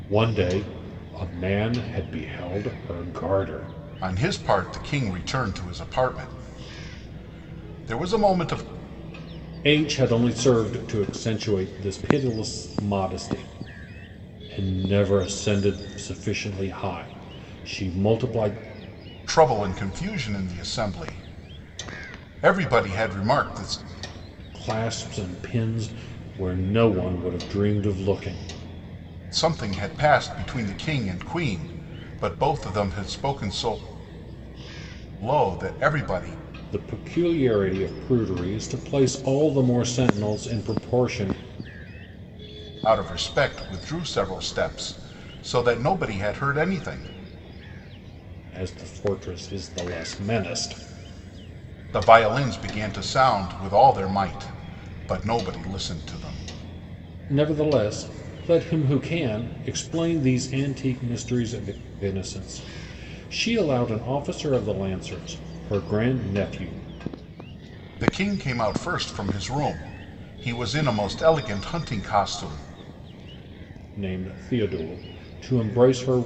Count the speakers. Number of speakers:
two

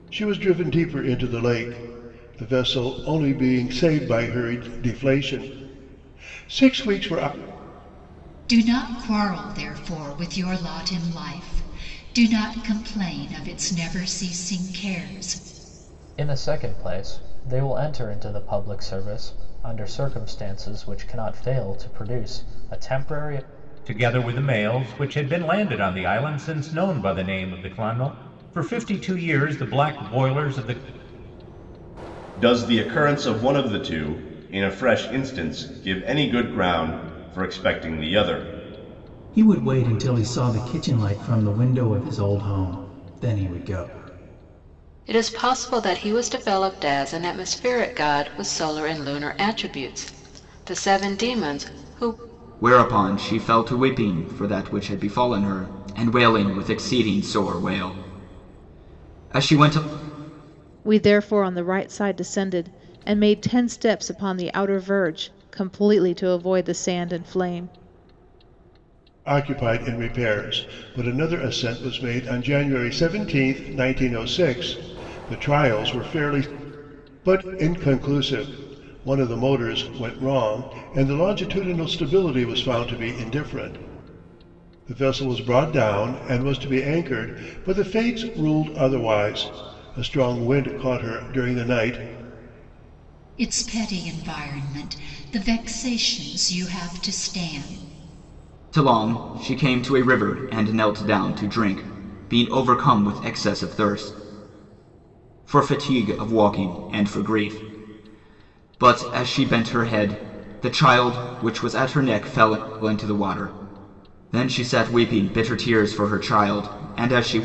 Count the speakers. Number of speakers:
nine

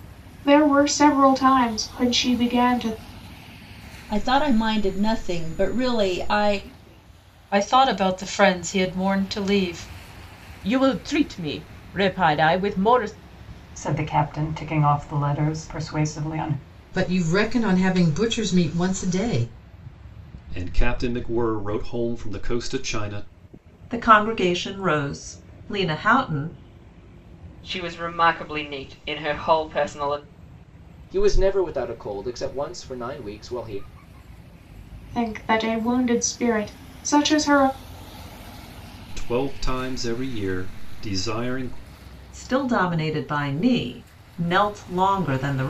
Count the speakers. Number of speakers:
ten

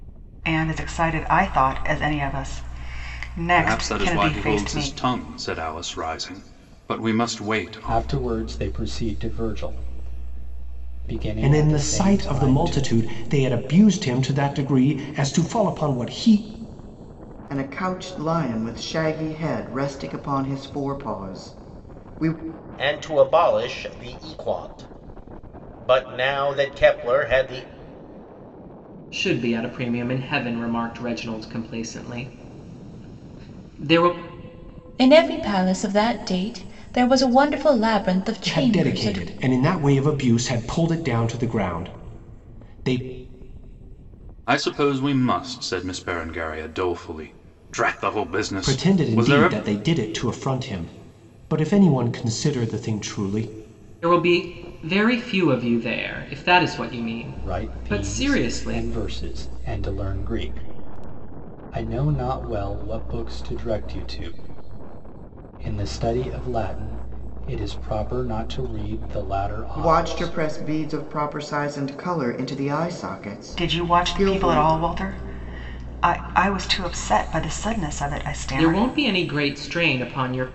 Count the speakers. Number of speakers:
eight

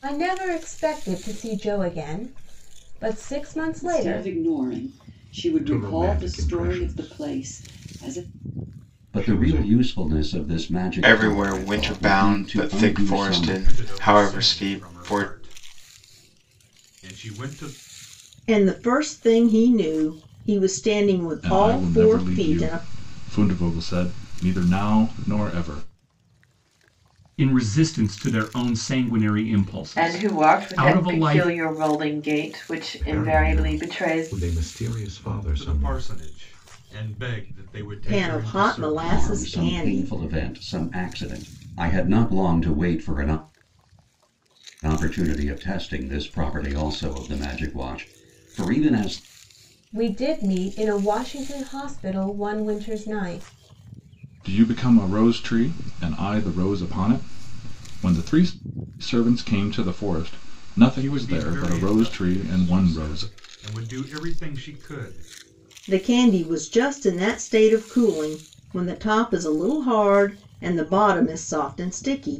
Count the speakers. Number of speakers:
ten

